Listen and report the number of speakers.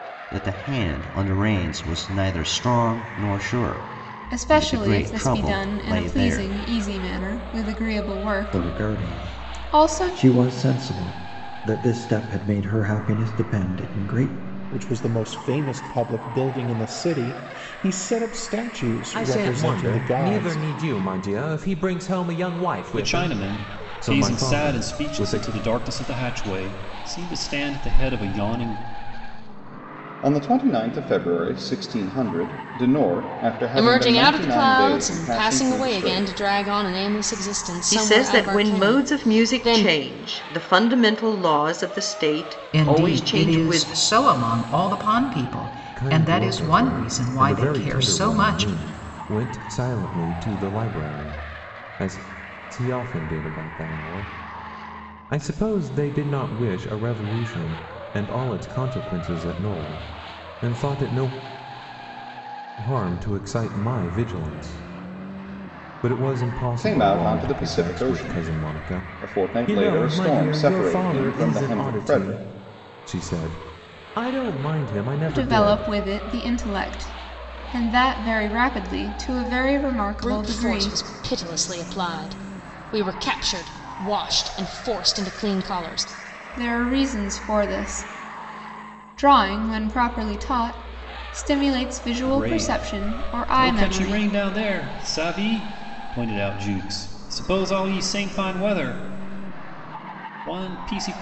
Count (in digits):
10